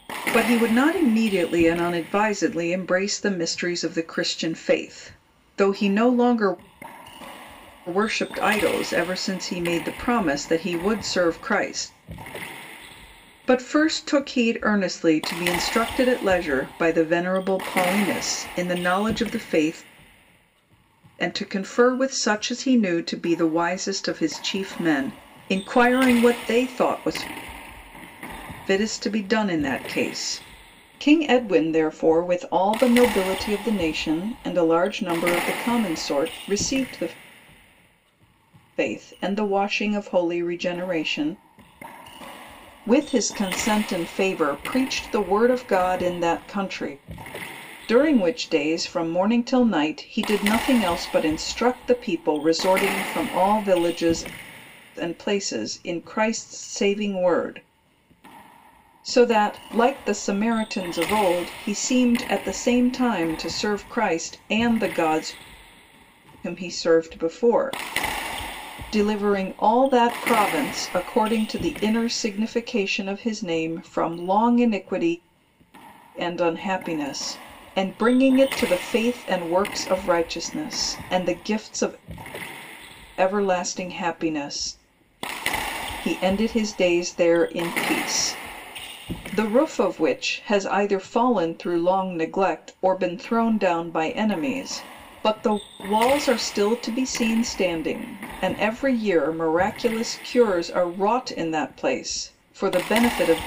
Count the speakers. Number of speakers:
1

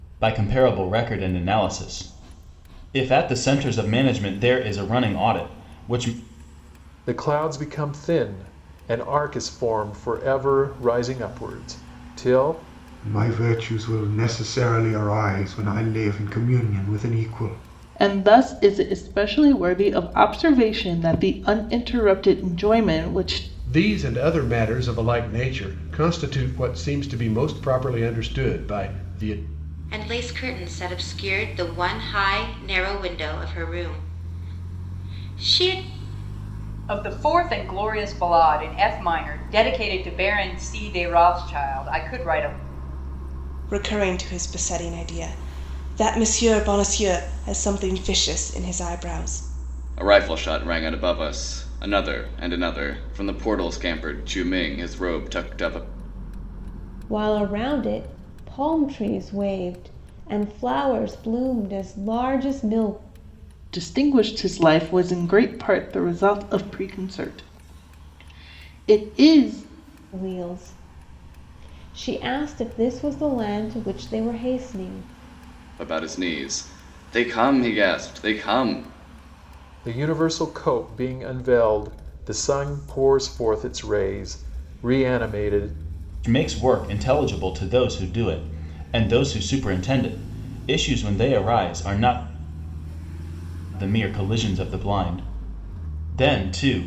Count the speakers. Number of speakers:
10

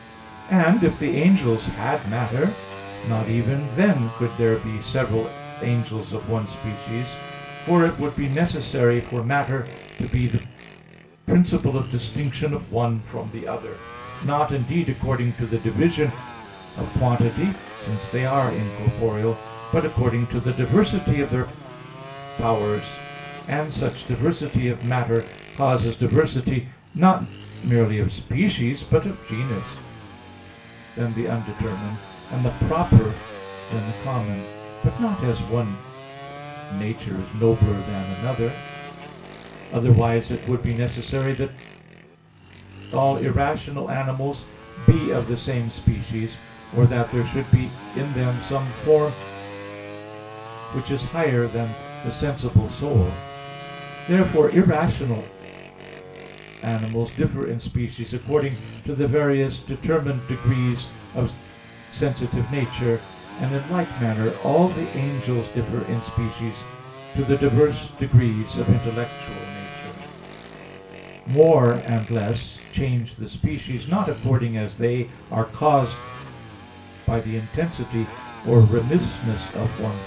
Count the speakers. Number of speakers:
1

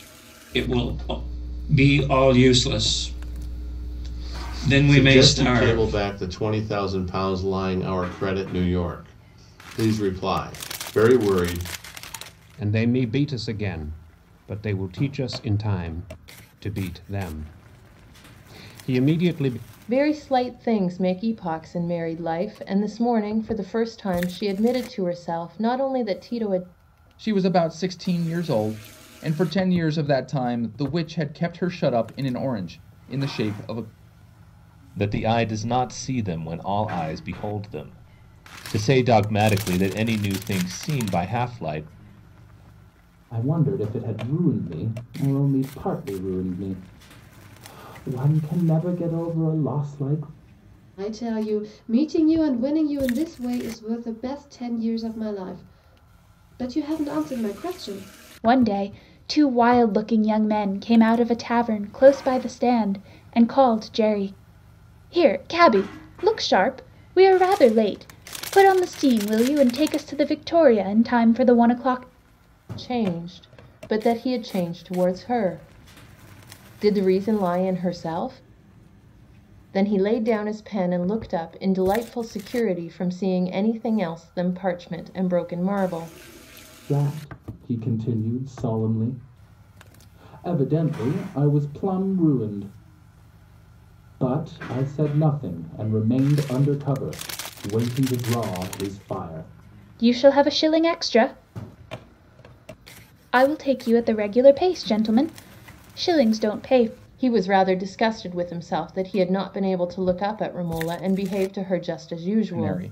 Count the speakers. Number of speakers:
9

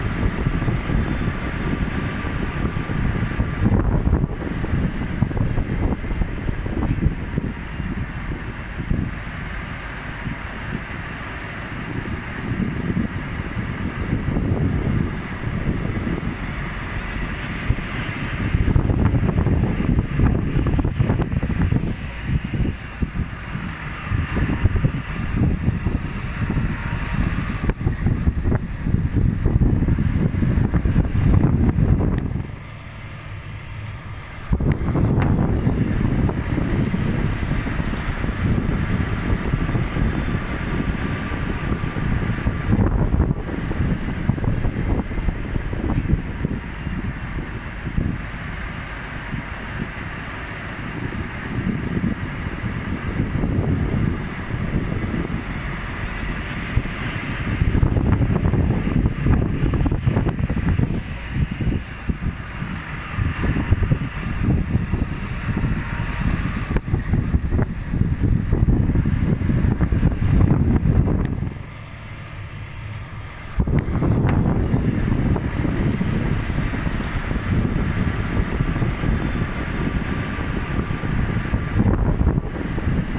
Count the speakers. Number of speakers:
0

